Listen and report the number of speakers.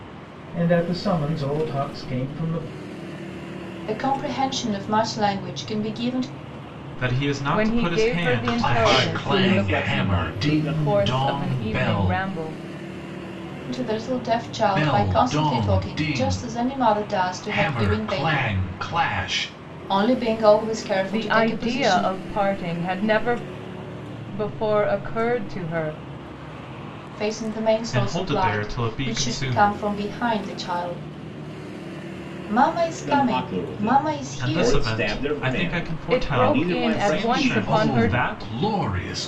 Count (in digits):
6